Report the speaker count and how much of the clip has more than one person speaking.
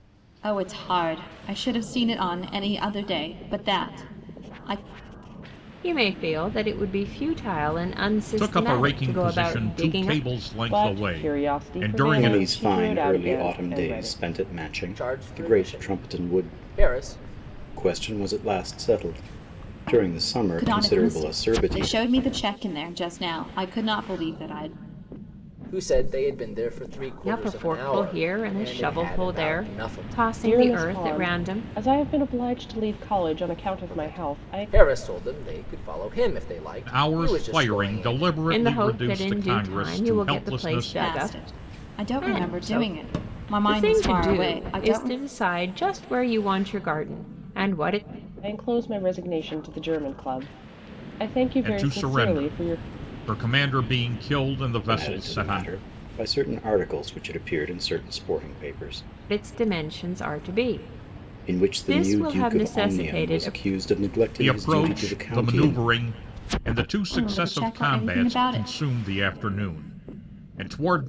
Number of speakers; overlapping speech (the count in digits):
6, about 40%